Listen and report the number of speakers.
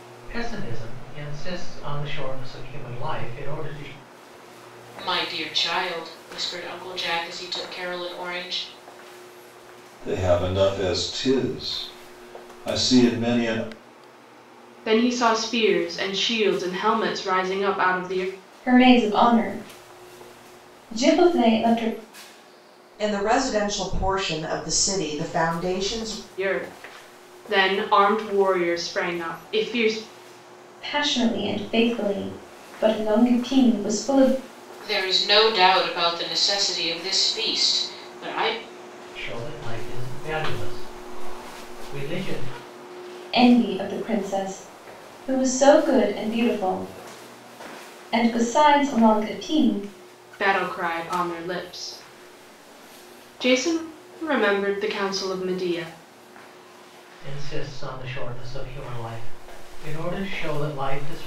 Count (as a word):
six